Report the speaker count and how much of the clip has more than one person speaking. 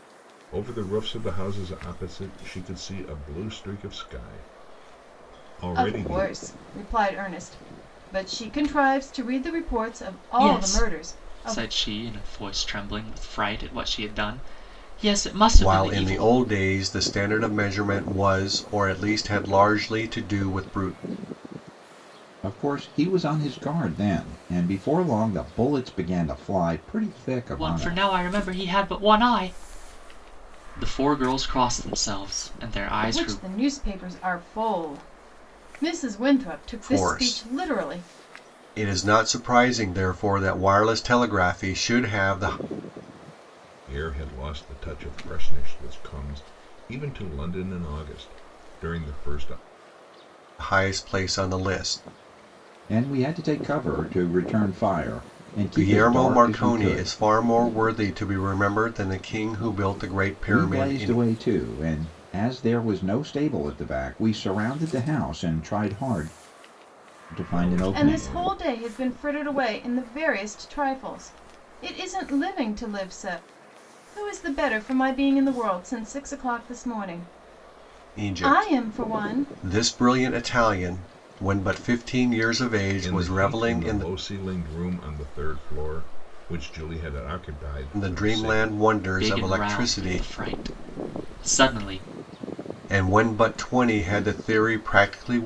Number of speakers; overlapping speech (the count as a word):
five, about 13%